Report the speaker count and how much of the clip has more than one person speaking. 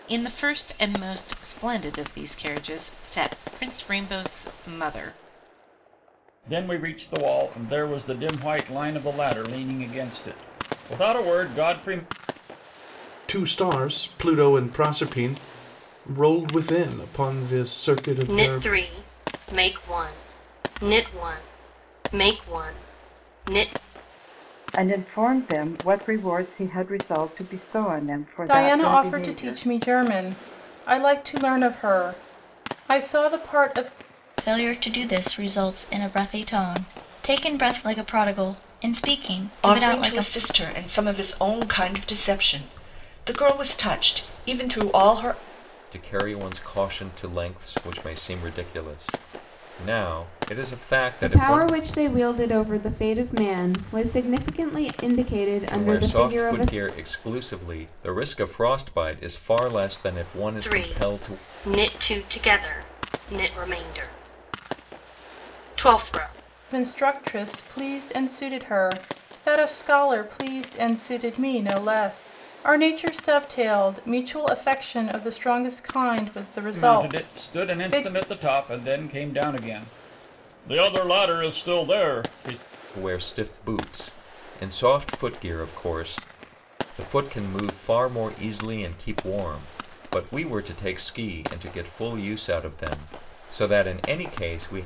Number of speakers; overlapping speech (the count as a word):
ten, about 7%